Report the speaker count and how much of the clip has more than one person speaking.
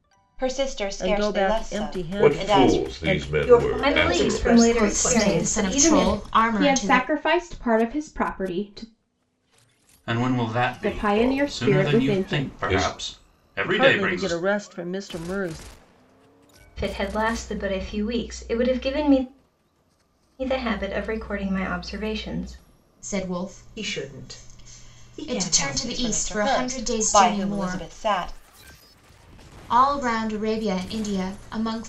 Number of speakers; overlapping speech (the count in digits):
8, about 40%